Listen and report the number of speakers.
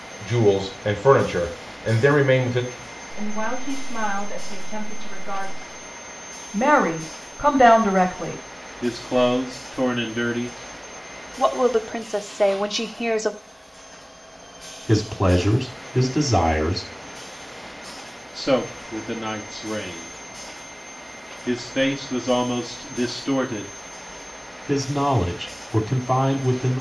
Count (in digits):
6